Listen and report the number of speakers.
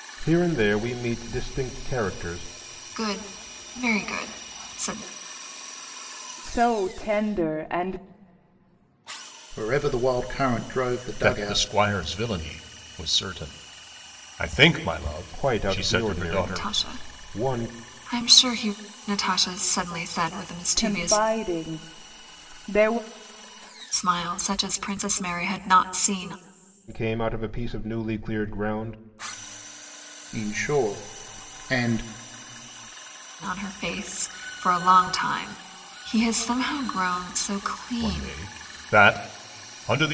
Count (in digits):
5